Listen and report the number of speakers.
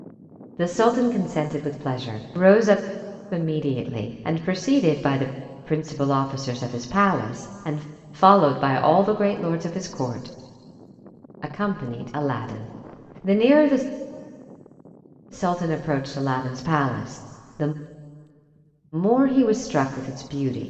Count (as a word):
one